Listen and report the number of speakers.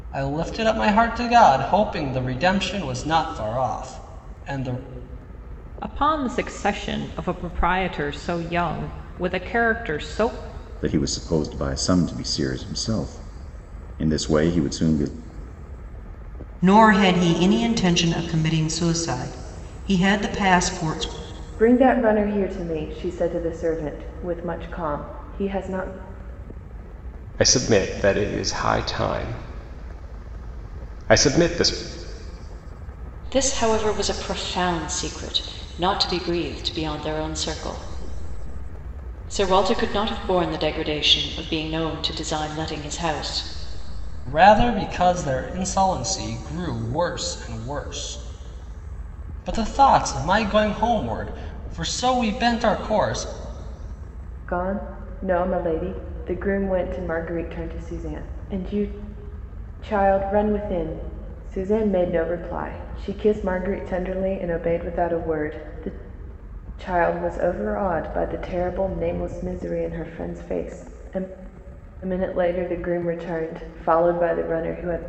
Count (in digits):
7